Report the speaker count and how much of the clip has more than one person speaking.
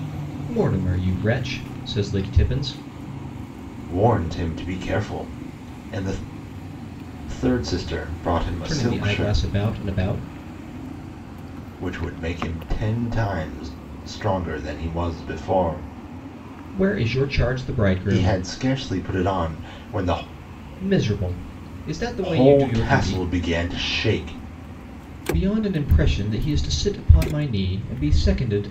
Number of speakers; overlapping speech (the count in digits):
2, about 8%